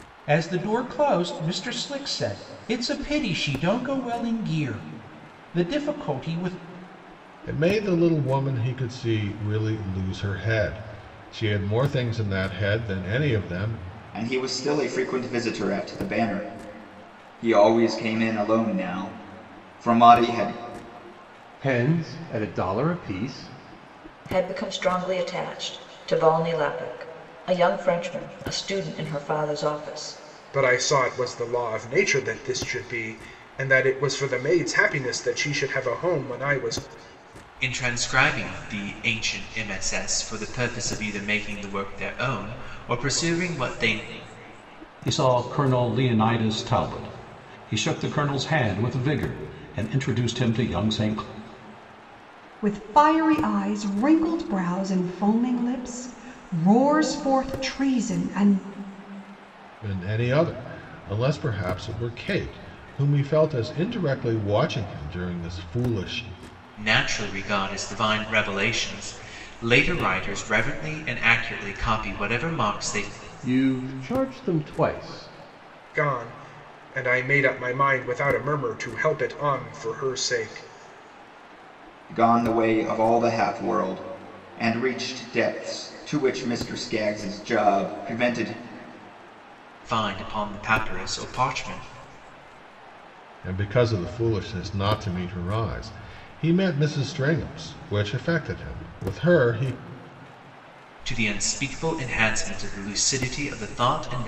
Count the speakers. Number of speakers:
nine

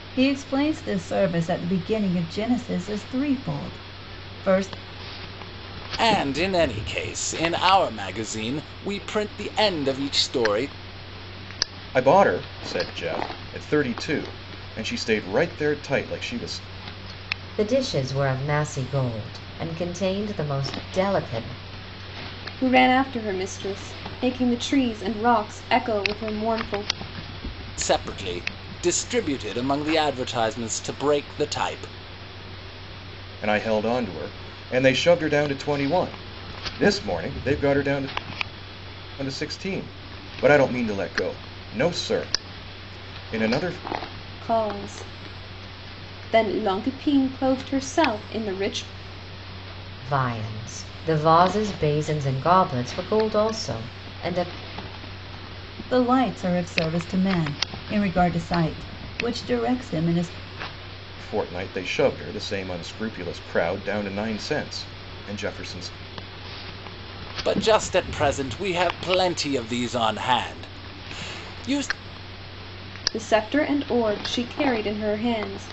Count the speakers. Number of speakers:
five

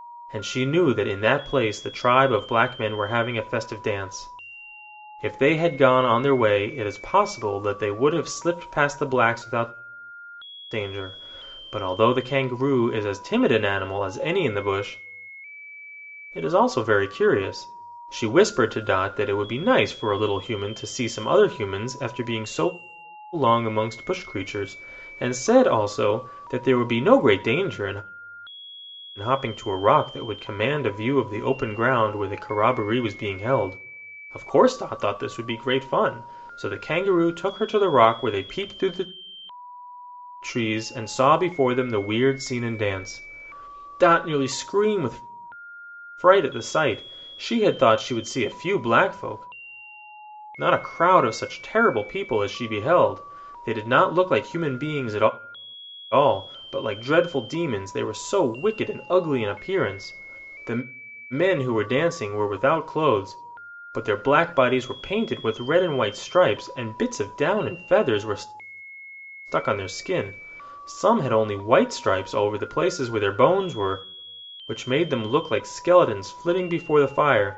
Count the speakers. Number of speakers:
one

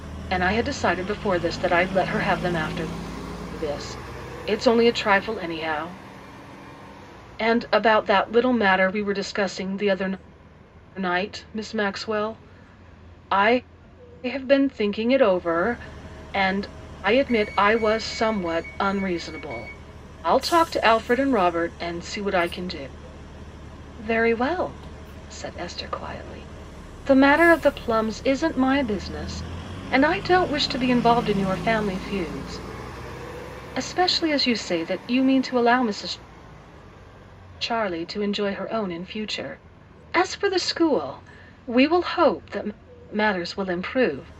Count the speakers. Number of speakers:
one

